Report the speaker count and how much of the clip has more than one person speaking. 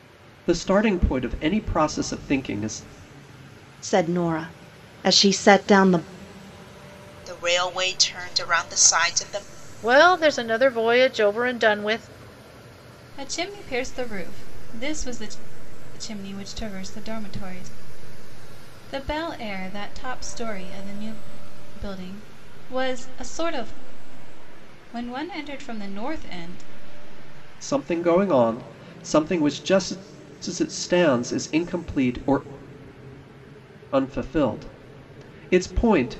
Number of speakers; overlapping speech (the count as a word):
five, no overlap